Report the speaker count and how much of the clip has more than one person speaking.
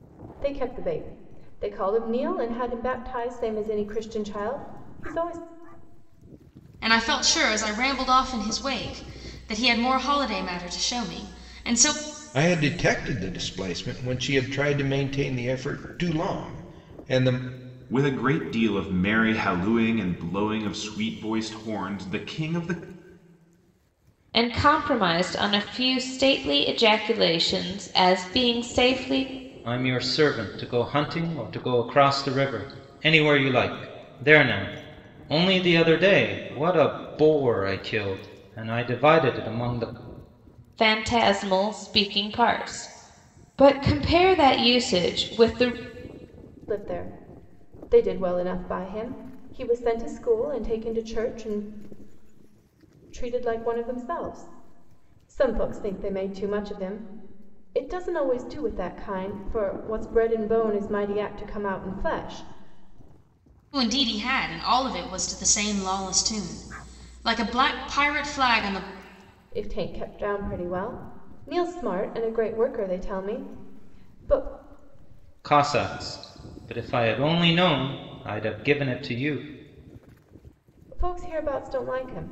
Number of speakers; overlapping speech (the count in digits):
6, no overlap